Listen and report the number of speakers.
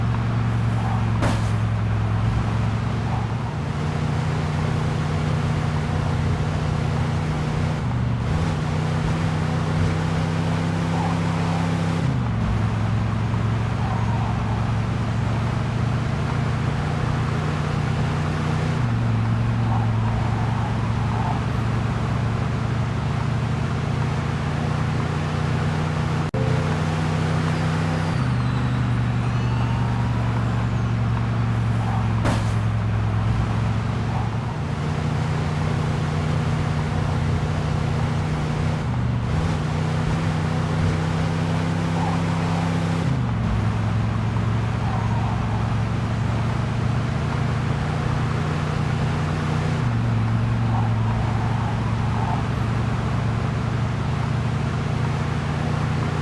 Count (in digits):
0